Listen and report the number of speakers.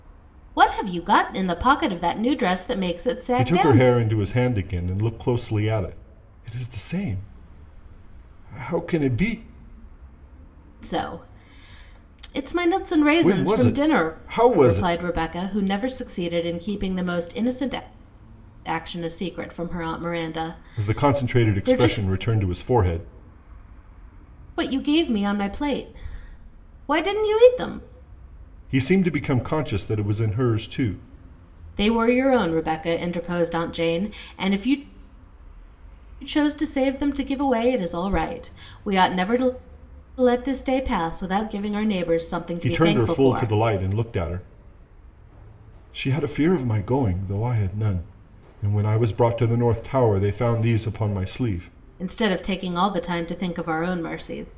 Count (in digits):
2